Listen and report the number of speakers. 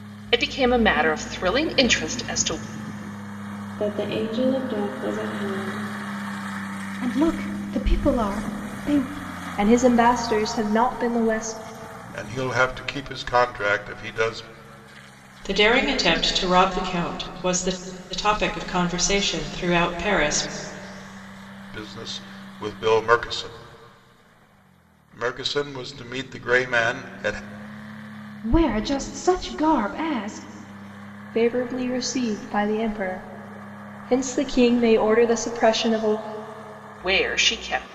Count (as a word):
six